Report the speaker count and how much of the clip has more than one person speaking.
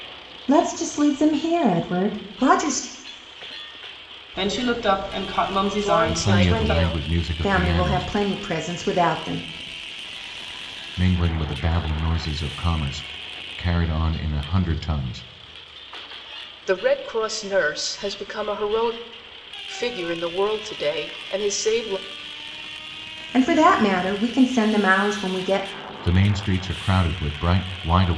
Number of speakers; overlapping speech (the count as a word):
four, about 7%